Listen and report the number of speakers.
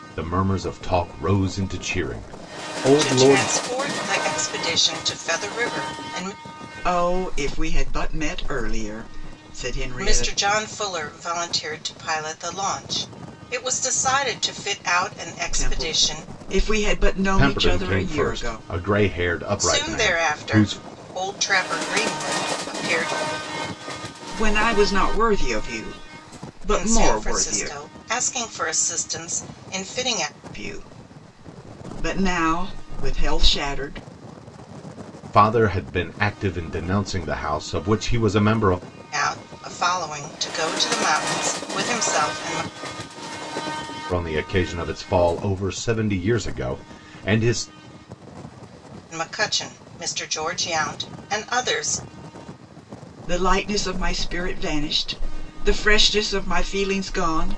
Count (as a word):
three